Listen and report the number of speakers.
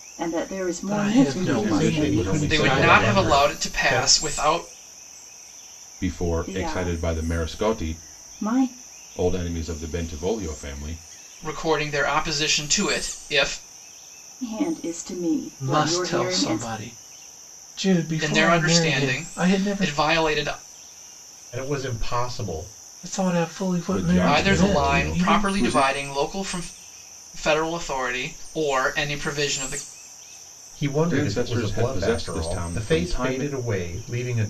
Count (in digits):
5